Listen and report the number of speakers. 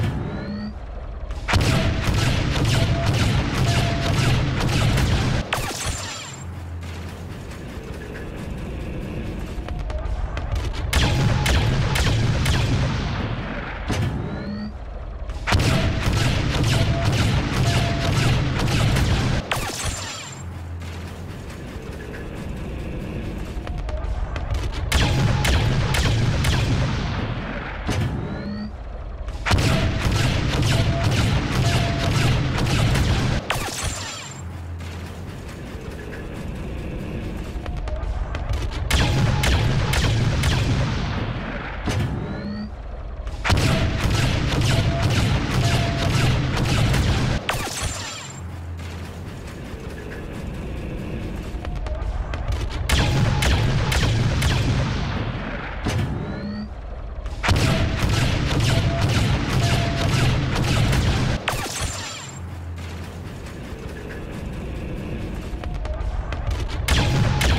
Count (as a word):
zero